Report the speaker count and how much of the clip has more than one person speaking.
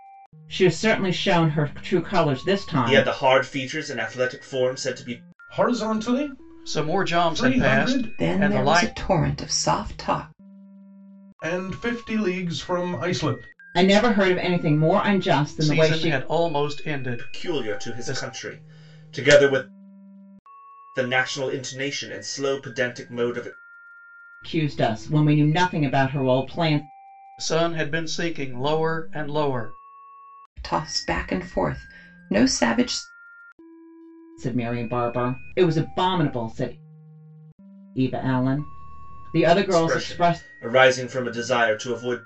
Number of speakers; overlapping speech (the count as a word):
five, about 13%